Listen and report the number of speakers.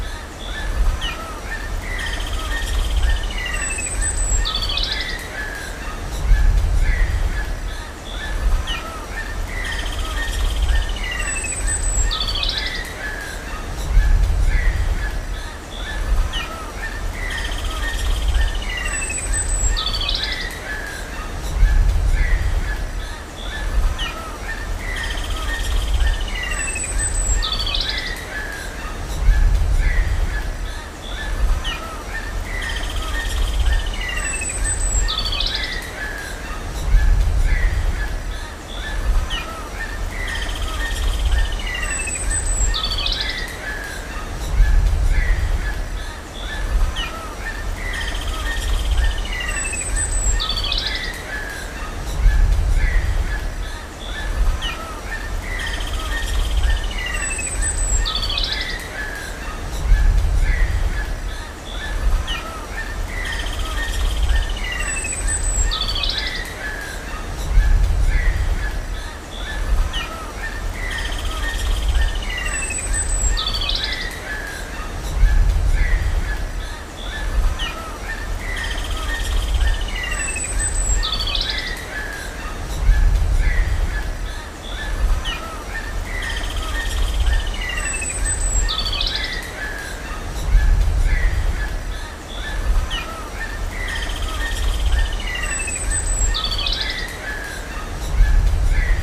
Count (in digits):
0